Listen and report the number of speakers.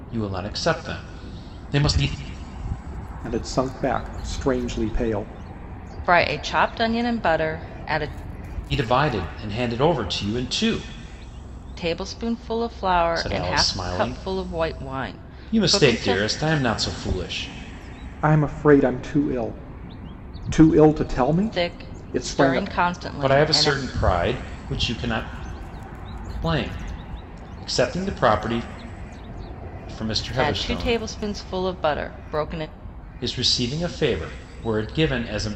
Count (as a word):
three